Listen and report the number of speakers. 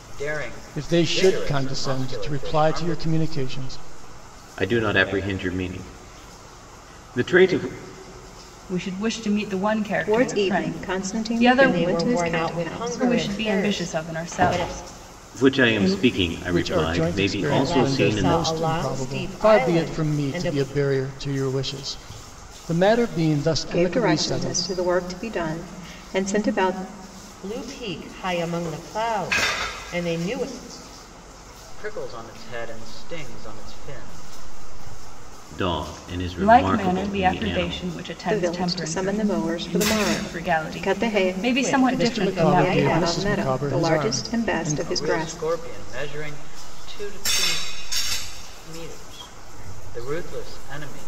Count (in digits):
6